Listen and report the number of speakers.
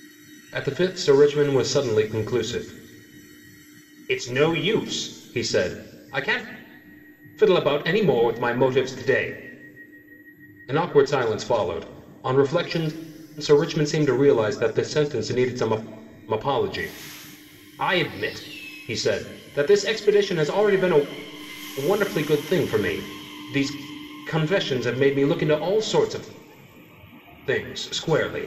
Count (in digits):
1